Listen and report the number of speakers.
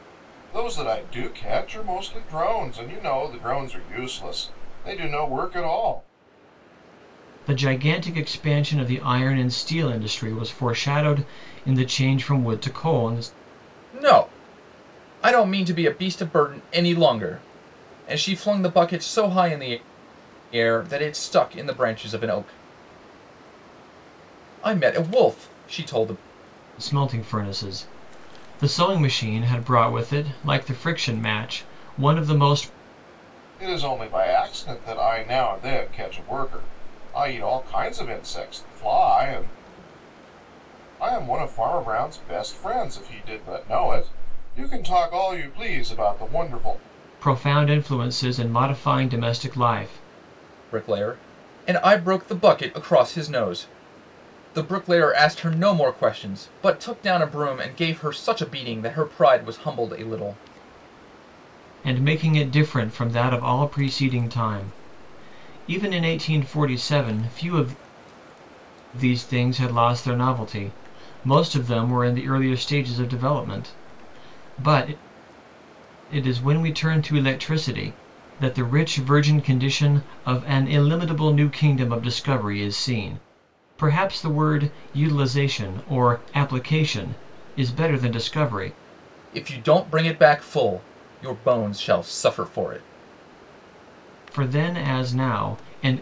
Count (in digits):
3